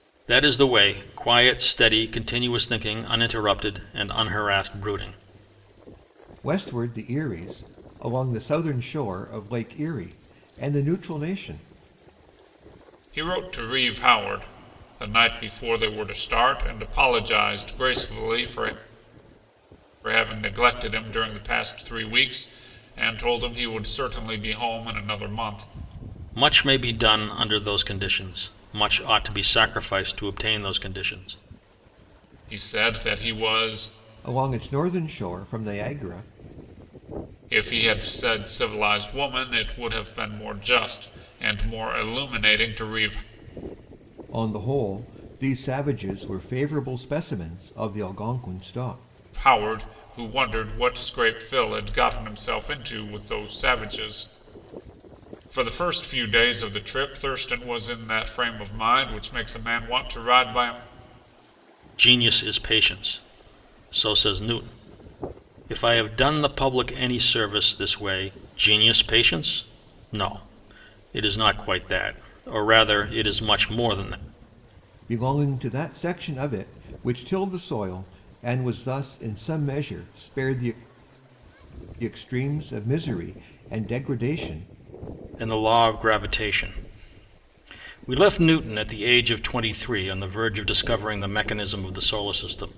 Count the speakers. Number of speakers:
three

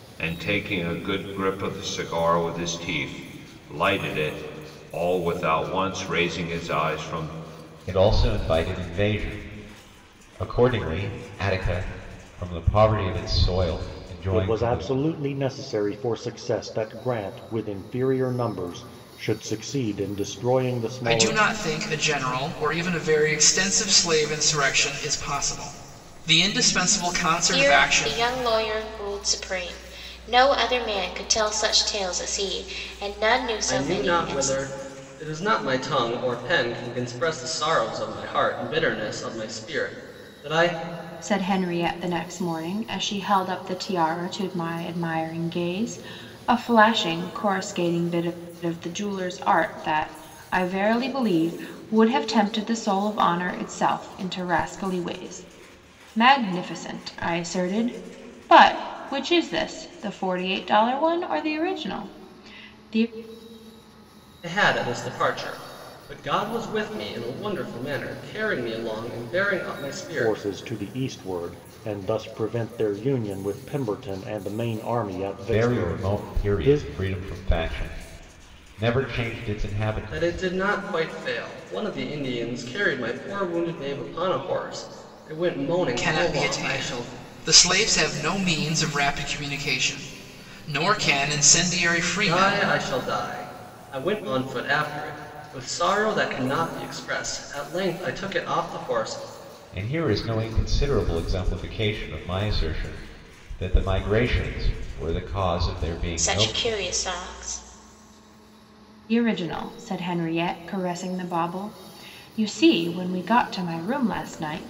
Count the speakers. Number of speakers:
seven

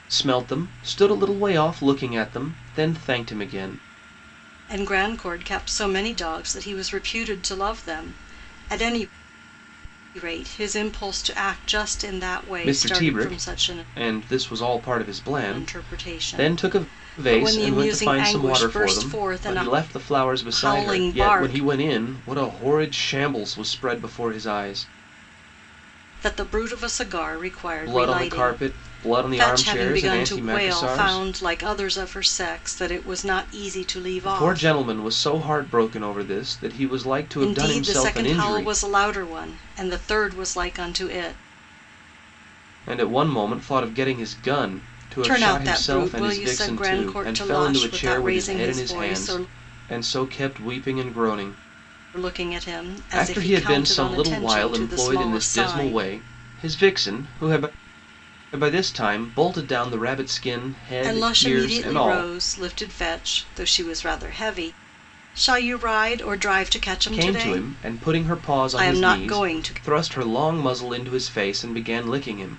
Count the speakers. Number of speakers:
two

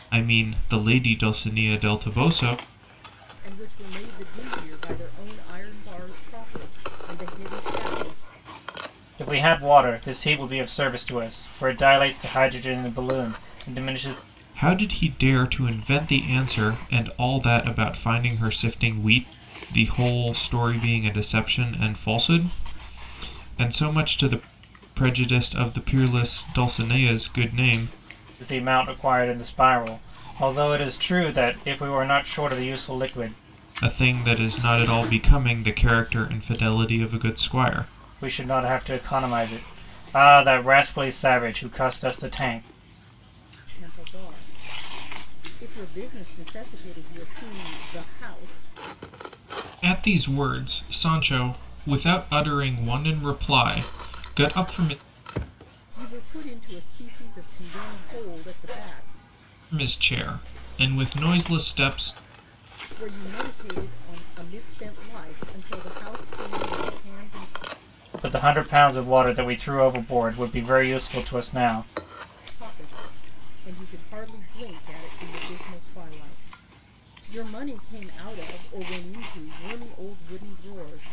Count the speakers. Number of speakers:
three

